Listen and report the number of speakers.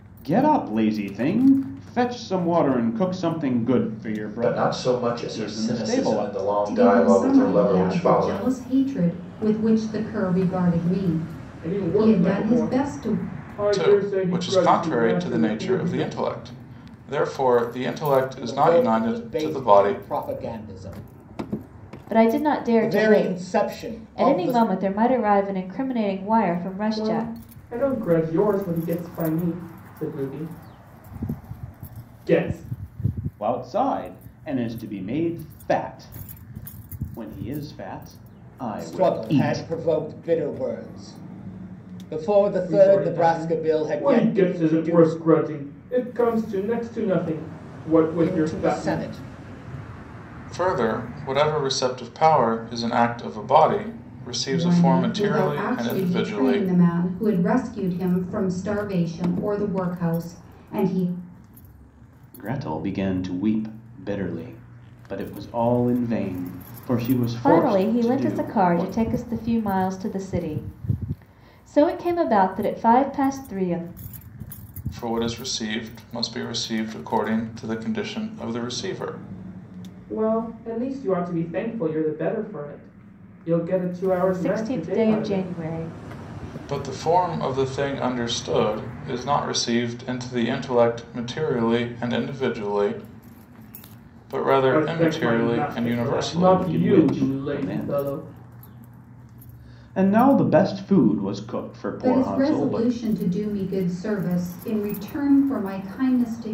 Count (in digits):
7